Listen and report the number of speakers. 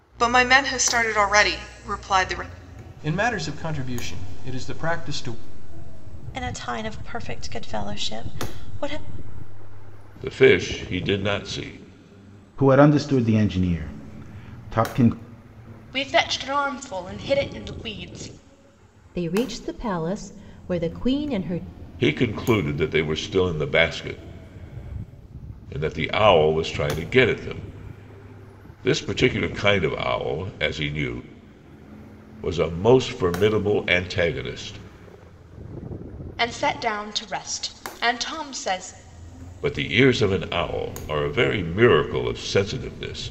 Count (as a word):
seven